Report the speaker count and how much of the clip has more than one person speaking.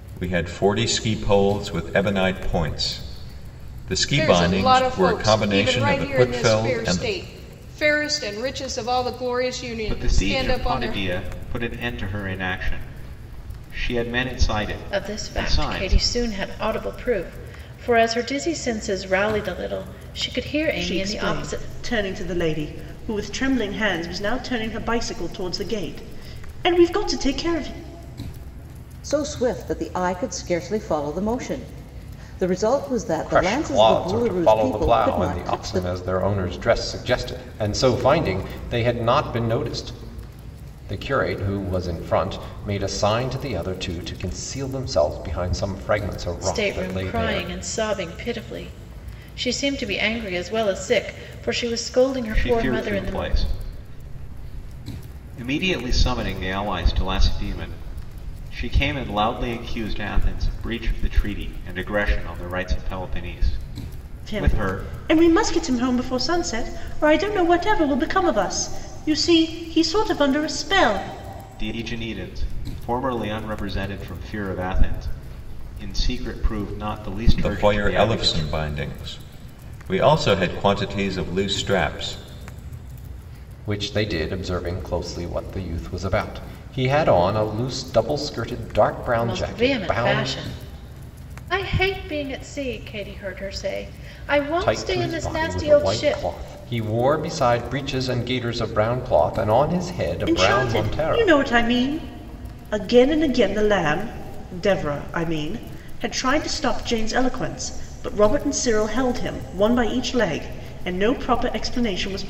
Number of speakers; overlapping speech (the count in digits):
7, about 15%